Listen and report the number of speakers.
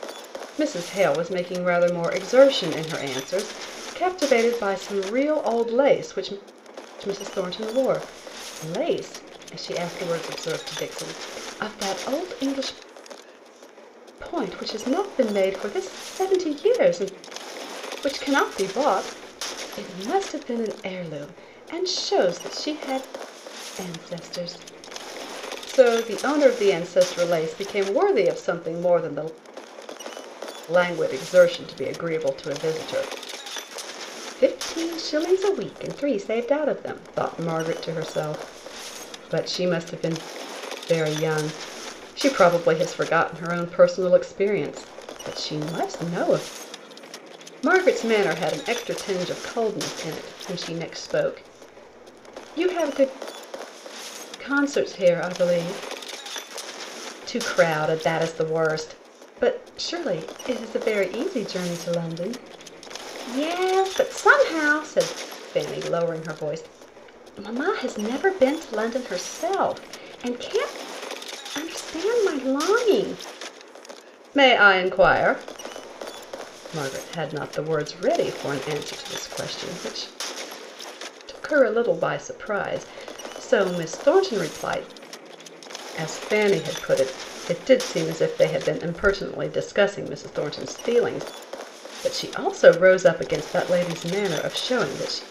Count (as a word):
one